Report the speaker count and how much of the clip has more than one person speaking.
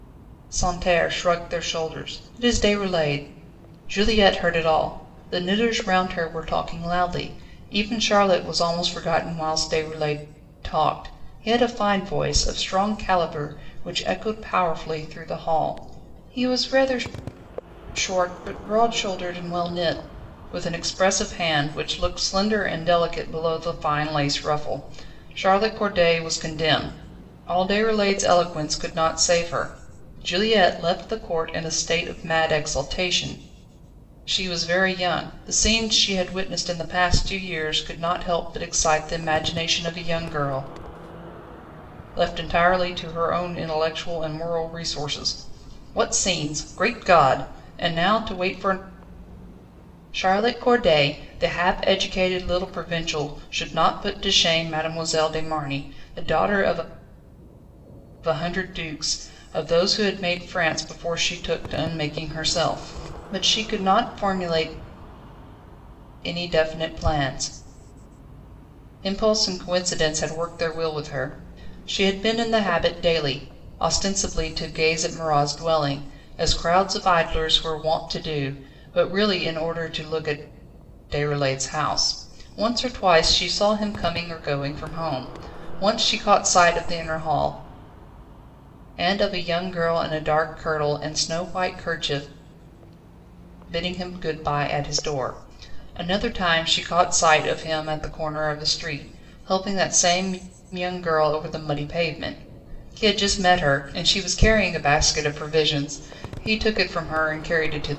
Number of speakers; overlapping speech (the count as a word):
one, no overlap